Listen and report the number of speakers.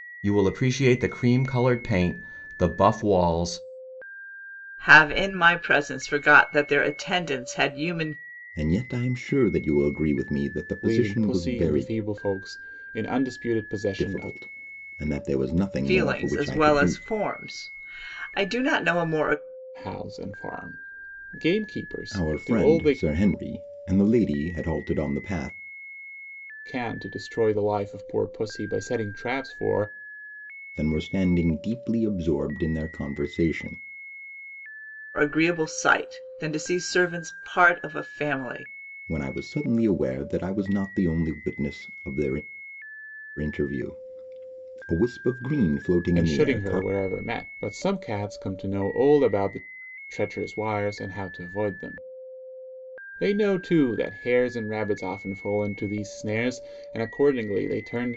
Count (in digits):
4